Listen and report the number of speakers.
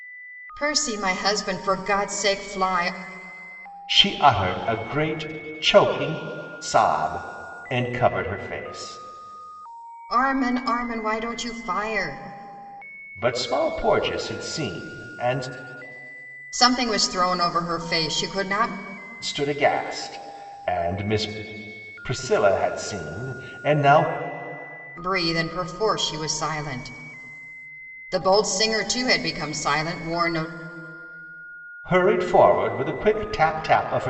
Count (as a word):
two